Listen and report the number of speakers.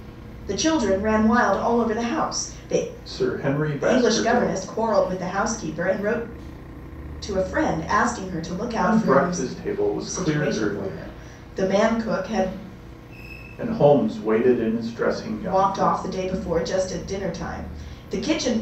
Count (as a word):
two